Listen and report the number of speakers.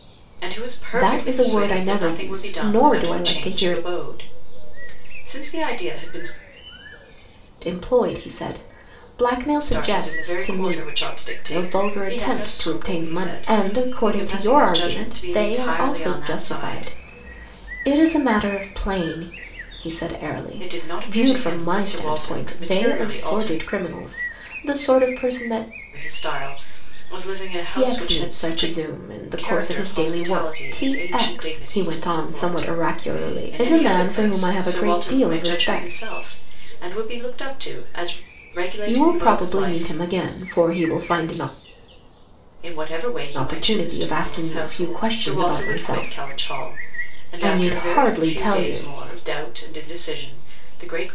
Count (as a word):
two